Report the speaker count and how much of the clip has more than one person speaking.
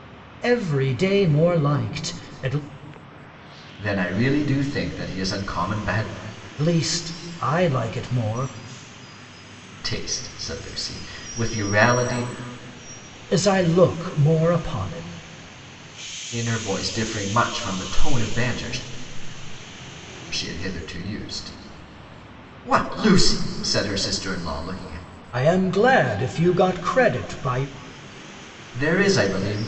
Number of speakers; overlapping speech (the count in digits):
2, no overlap